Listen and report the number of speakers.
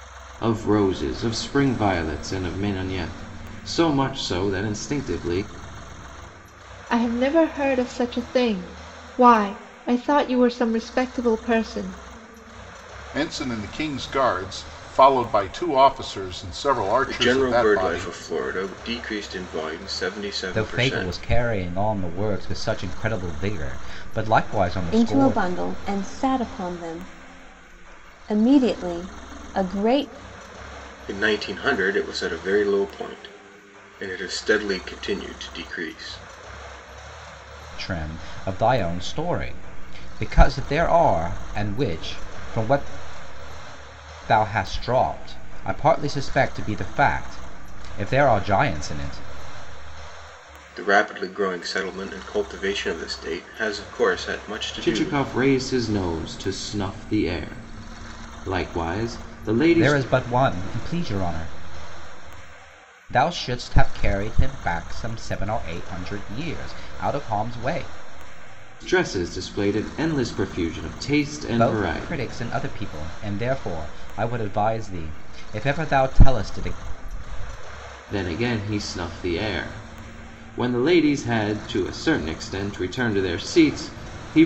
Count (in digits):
6